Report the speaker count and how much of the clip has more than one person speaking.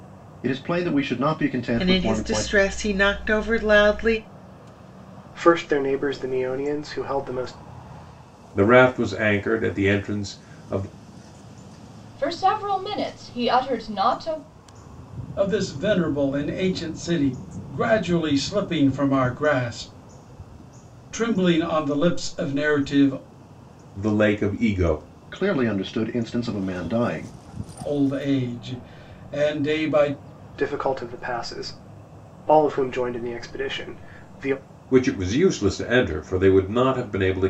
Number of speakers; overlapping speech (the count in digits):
6, about 2%